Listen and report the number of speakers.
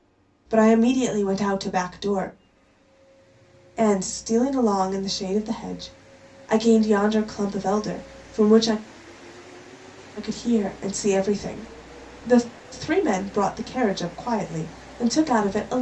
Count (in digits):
1